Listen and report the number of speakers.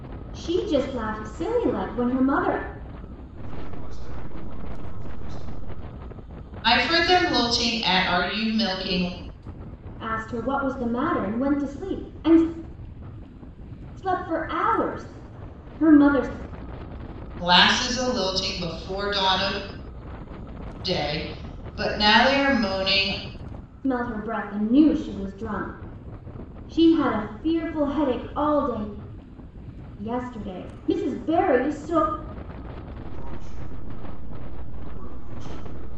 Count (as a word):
three